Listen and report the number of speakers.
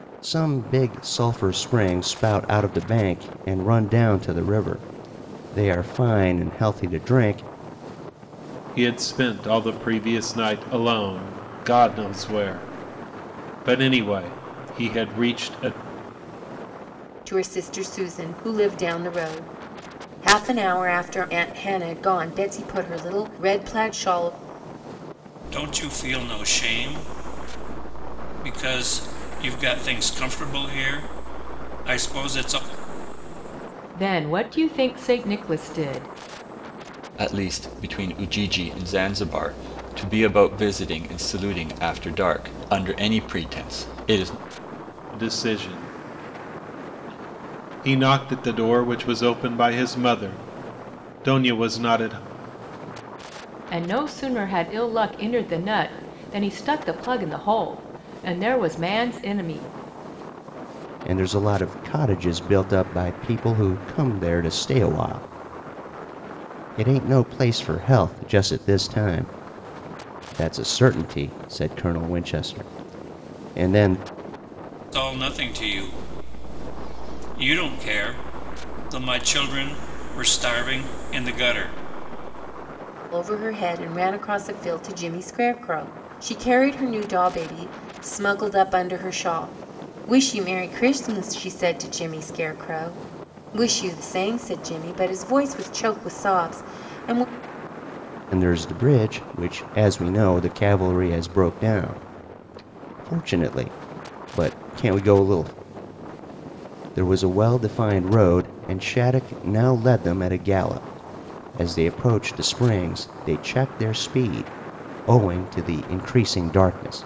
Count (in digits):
6